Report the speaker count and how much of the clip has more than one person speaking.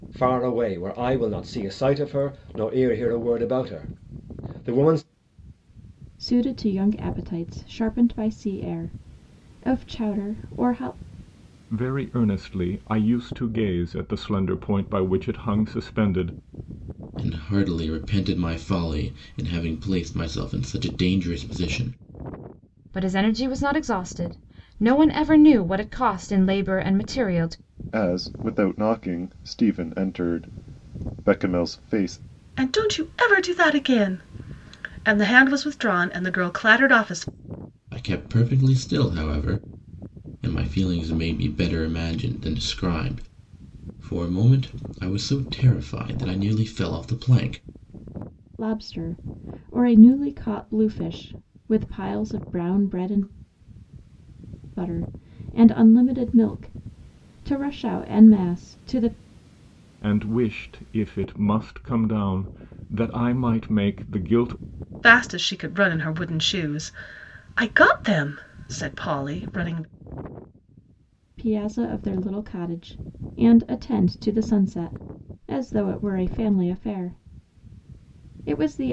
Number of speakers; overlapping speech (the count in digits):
7, no overlap